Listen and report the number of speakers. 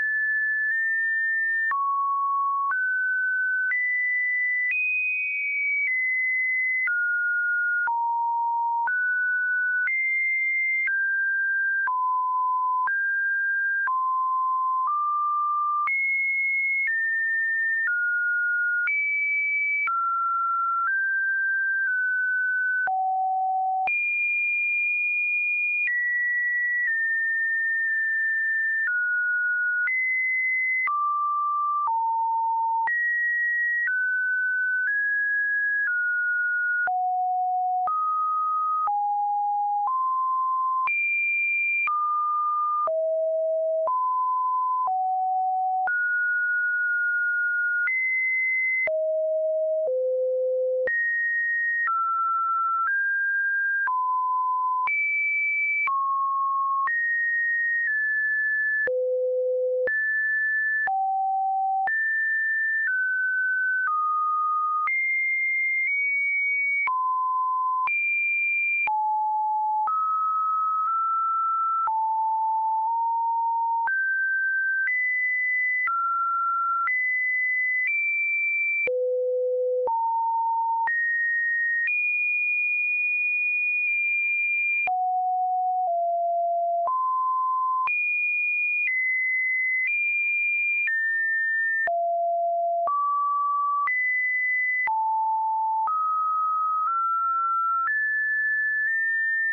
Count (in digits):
0